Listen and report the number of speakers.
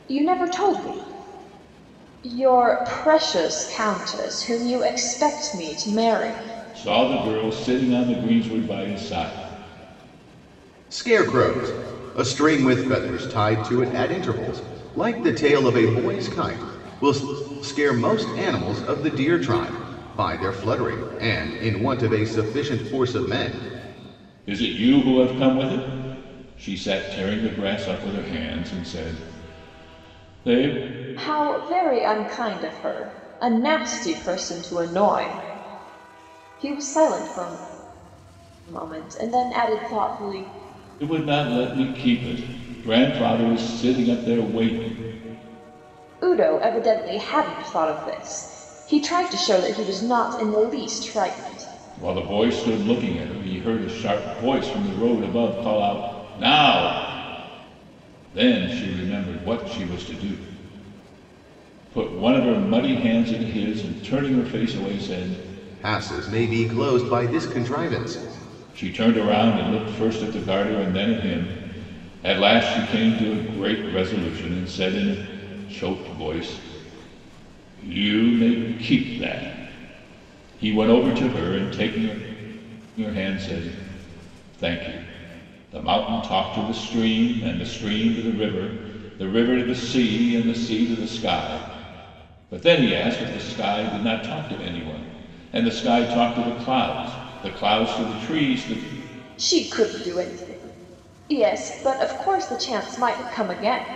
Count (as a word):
three